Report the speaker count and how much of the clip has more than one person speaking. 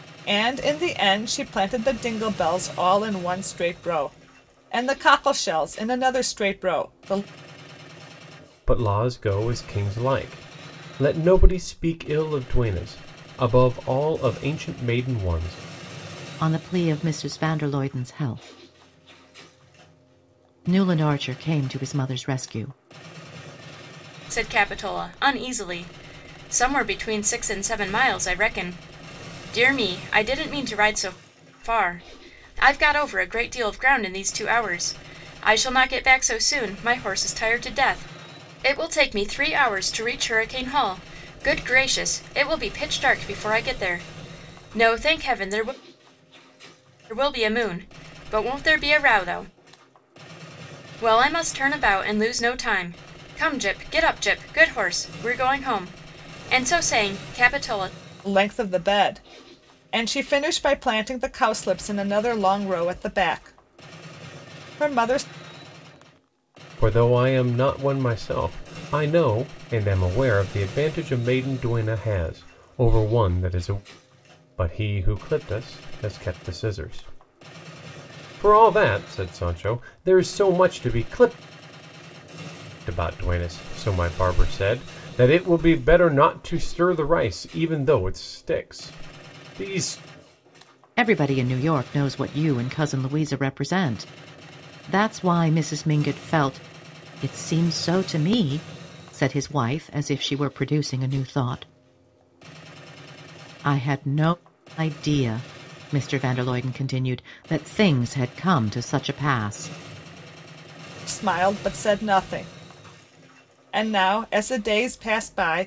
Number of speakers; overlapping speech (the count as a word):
four, no overlap